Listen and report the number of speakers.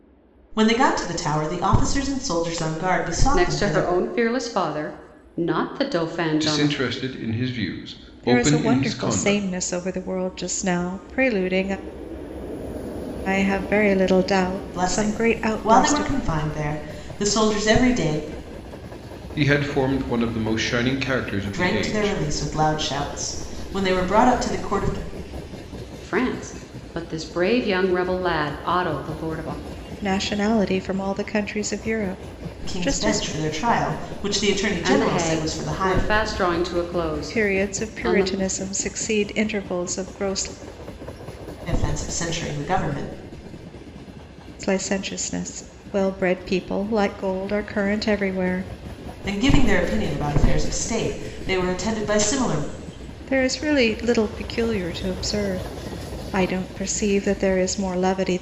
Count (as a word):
four